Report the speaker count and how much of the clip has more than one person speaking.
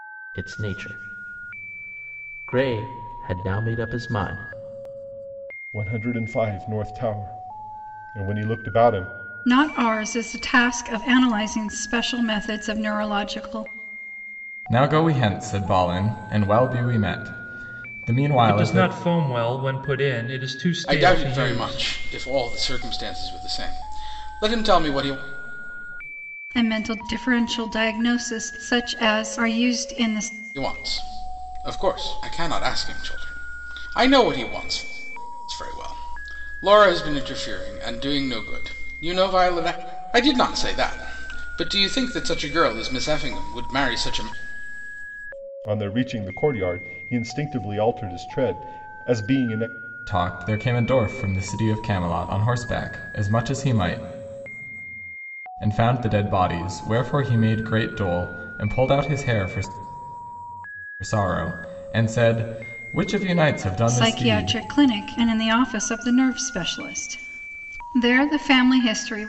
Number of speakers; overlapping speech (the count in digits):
6, about 3%